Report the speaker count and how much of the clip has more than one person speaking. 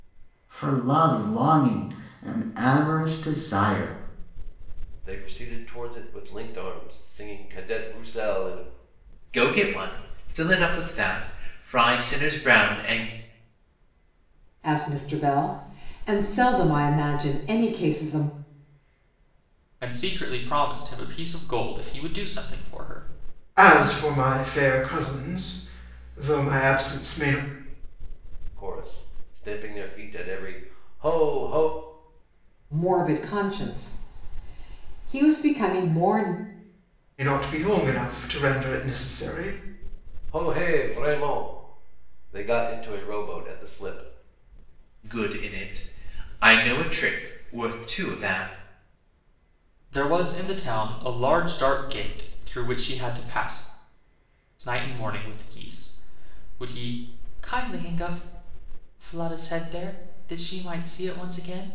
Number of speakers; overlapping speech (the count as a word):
six, no overlap